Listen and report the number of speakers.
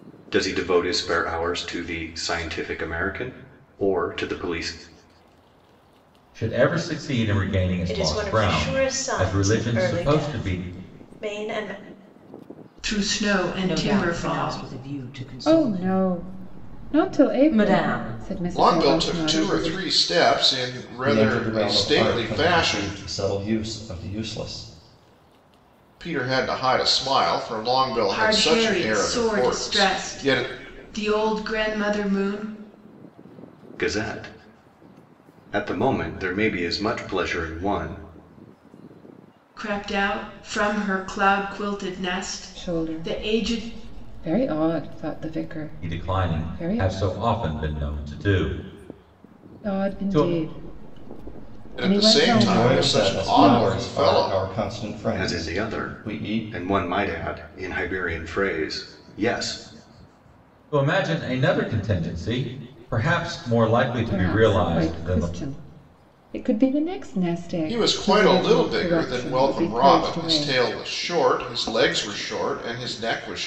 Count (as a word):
eight